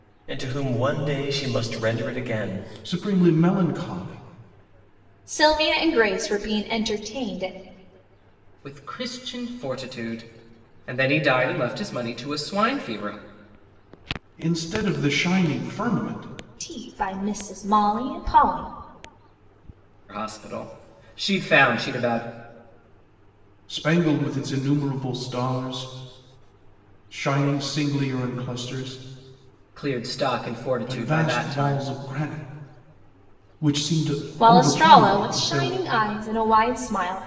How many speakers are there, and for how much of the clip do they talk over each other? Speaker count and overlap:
4, about 7%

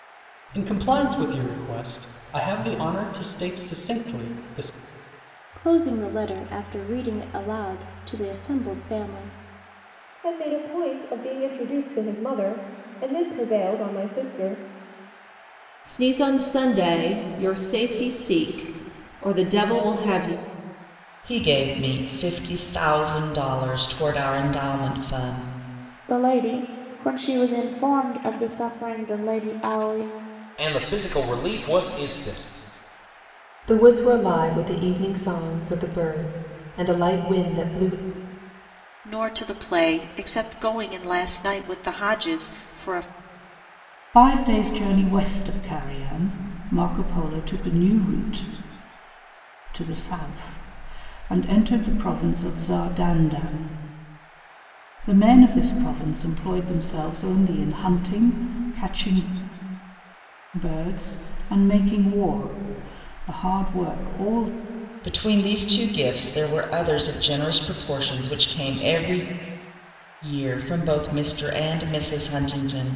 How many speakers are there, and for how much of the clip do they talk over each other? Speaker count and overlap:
10, no overlap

